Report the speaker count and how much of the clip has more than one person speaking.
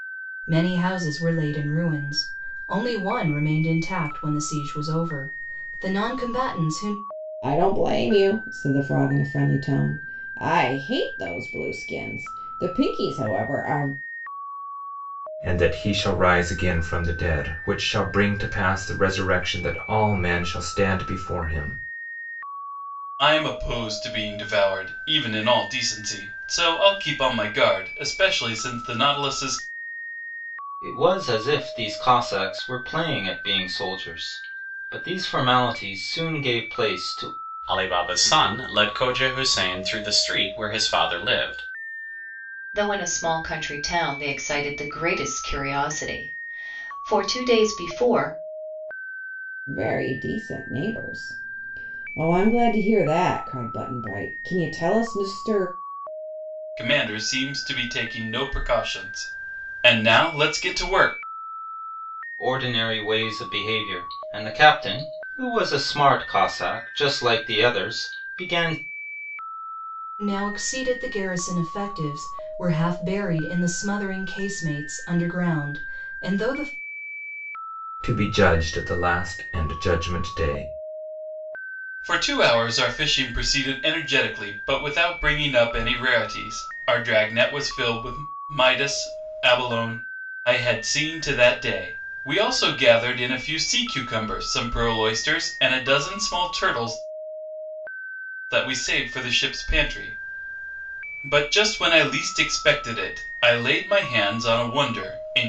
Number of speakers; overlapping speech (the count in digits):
7, no overlap